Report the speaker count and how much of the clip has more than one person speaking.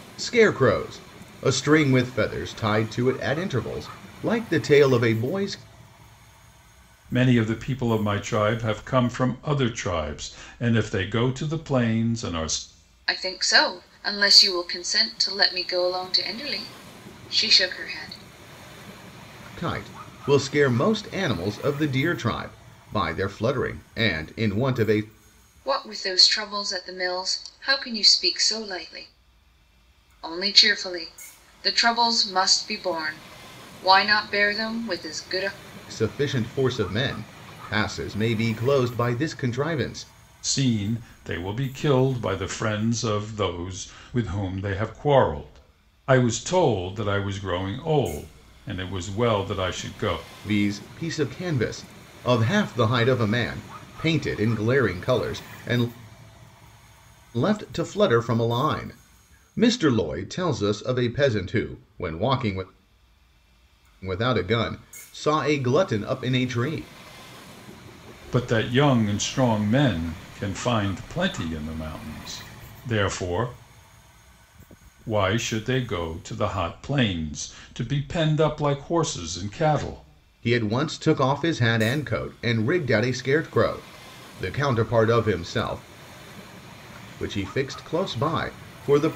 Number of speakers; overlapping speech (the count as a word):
three, no overlap